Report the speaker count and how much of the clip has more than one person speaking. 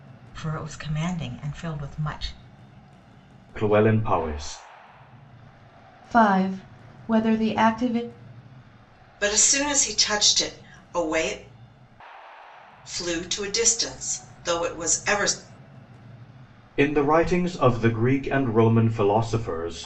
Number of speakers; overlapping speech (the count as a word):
four, no overlap